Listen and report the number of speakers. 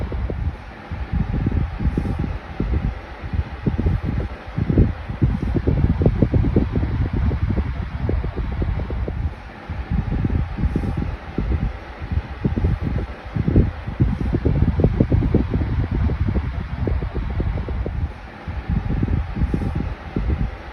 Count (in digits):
0